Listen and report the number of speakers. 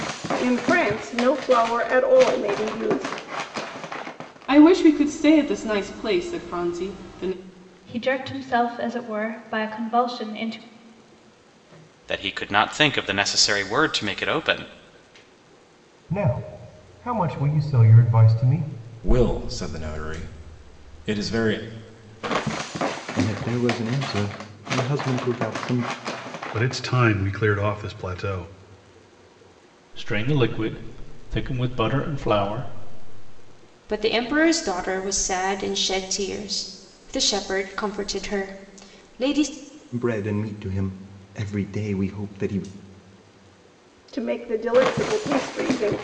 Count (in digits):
10